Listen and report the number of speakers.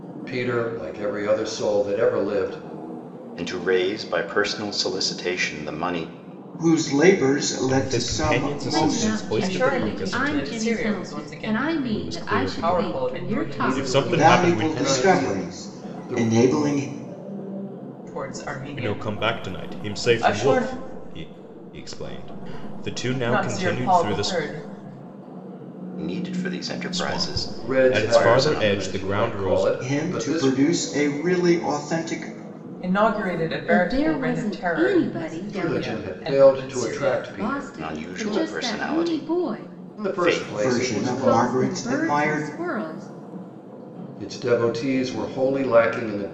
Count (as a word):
six